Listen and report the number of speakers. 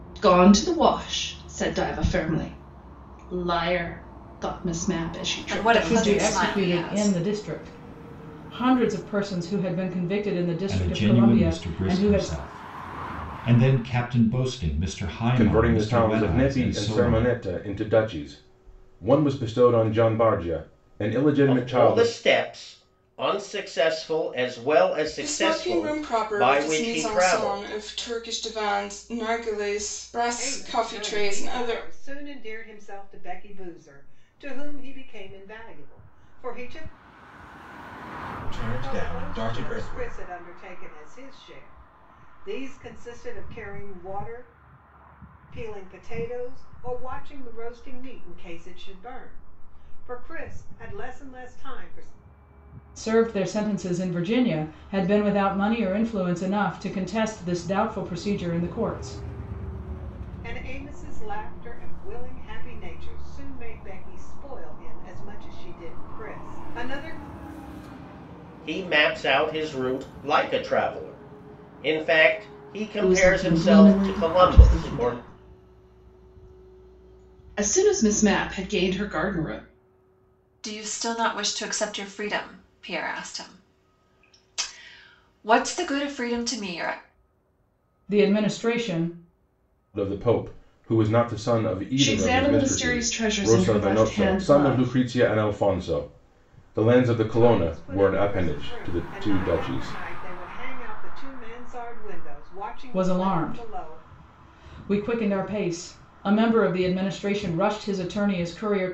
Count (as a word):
nine